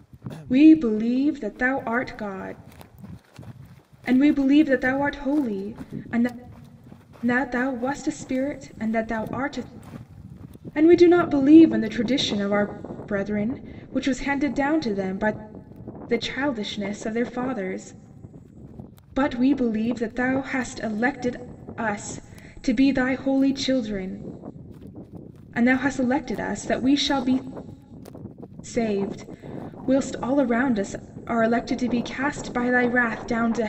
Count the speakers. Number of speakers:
1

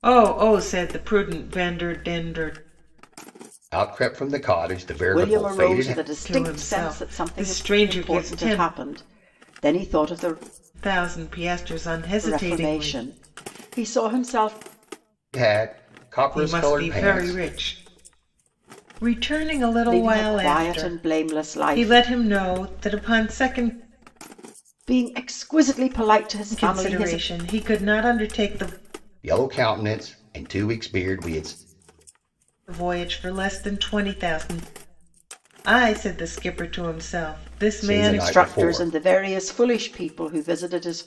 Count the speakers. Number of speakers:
3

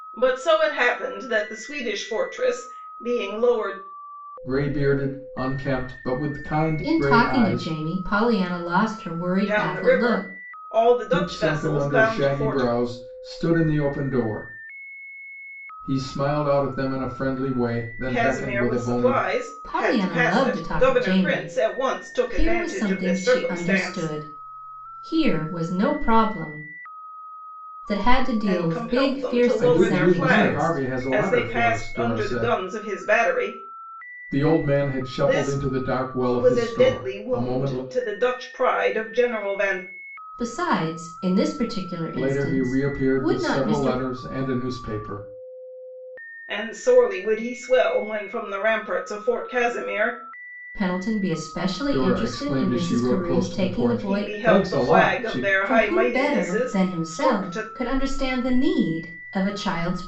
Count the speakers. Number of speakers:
3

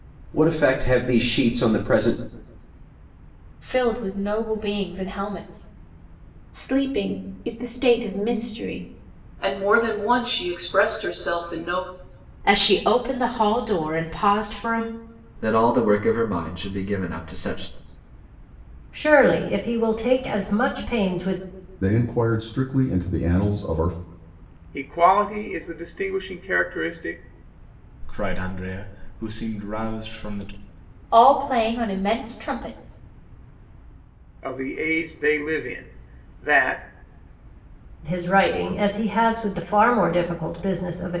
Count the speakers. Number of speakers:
10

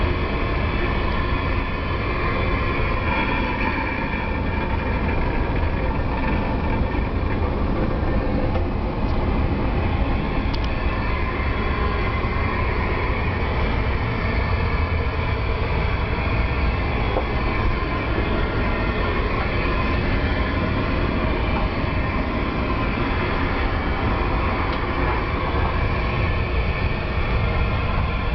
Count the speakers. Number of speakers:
0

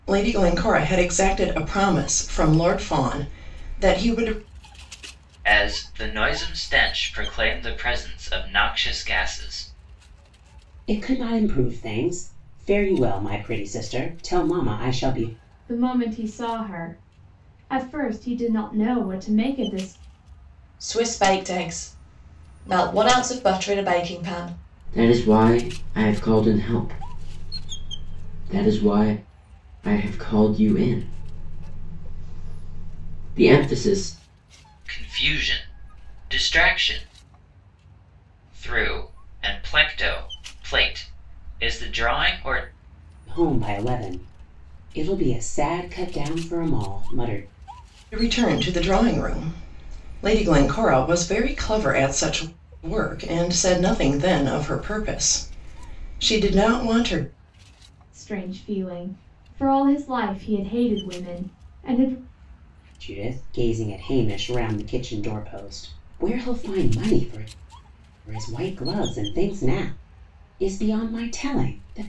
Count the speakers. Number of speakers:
6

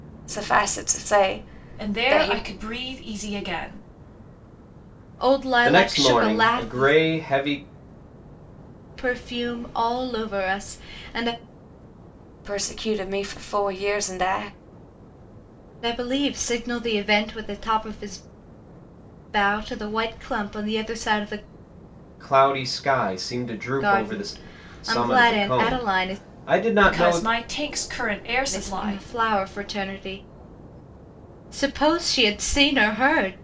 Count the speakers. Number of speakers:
4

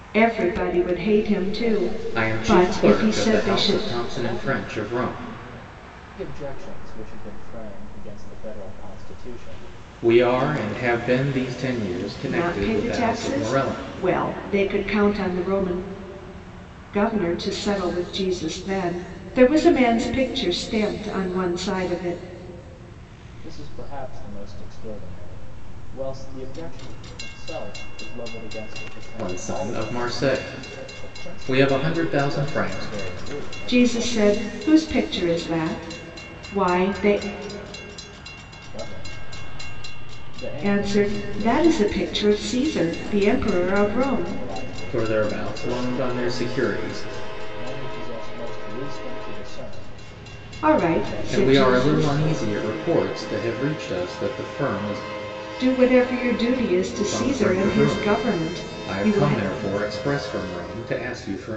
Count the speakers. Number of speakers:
3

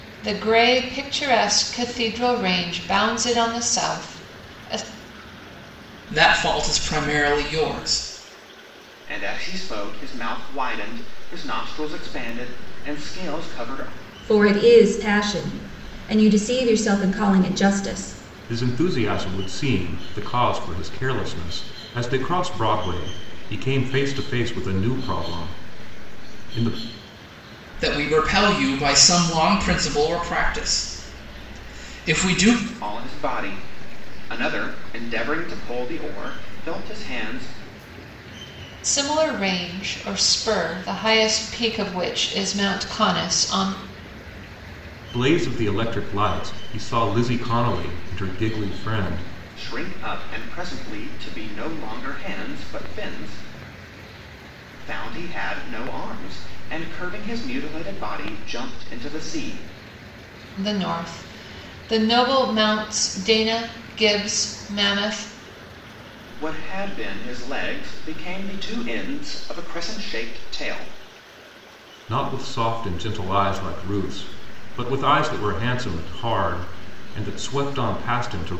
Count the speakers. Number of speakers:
5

